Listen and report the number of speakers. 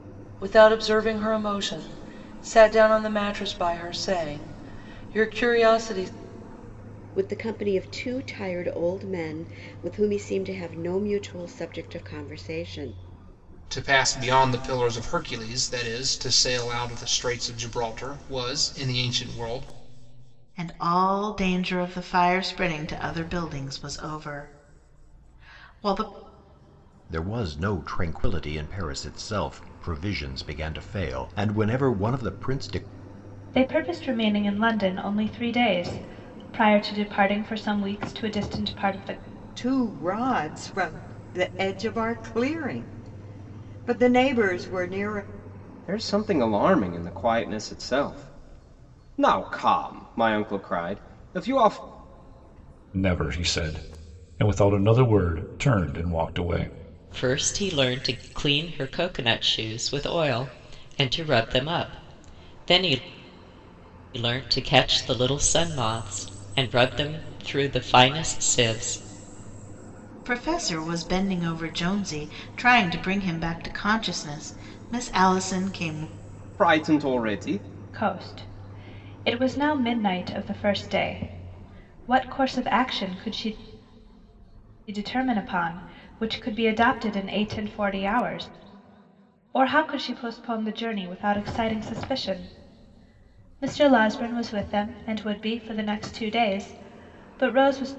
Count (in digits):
10